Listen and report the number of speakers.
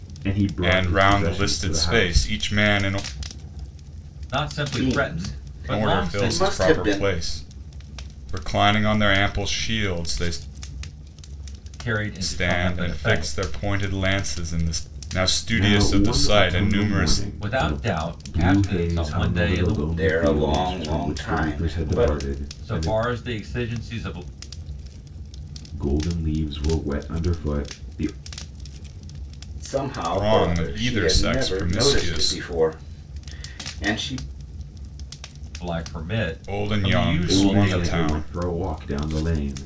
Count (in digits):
4